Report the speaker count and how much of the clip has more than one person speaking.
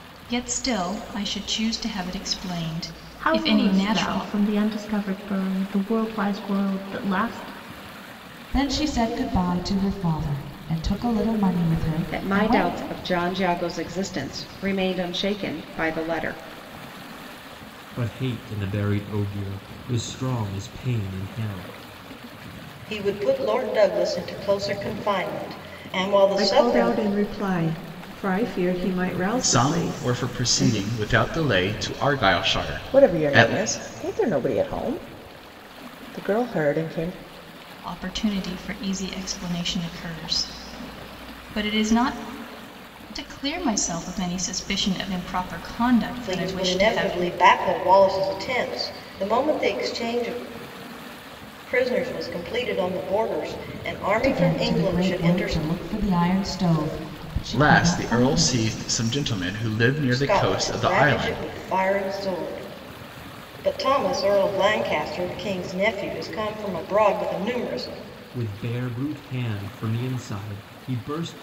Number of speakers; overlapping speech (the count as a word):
nine, about 13%